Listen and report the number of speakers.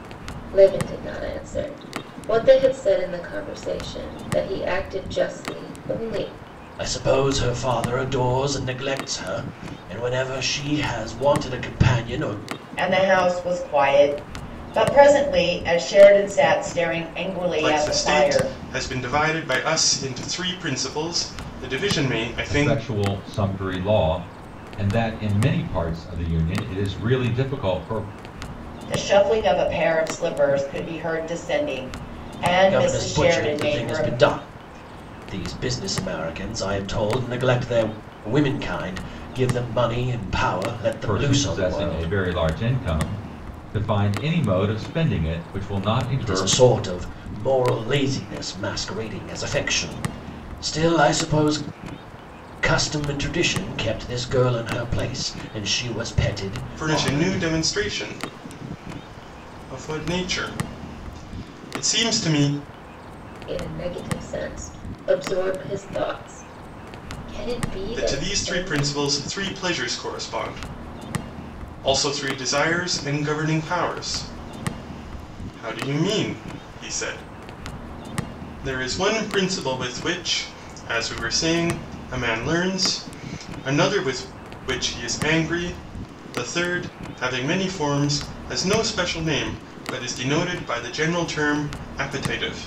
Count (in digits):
5